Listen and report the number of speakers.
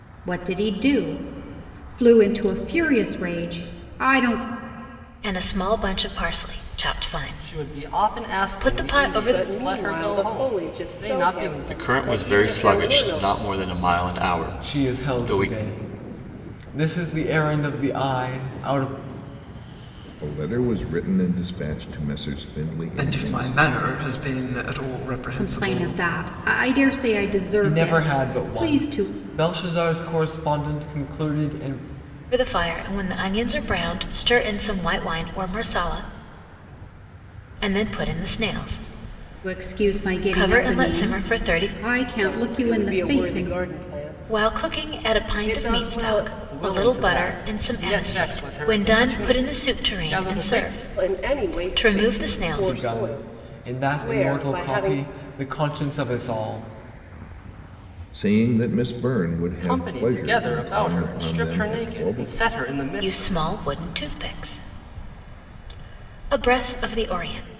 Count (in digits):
8